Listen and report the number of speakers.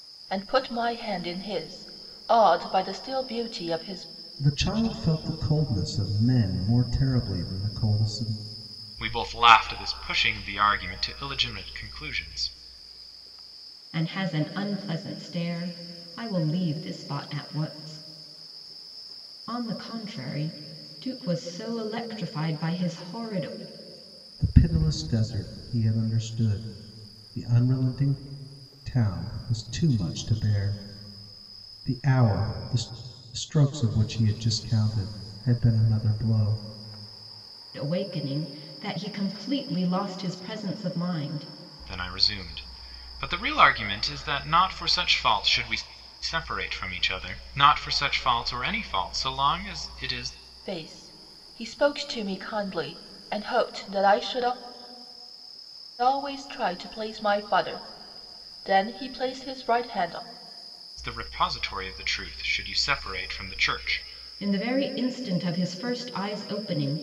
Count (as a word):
four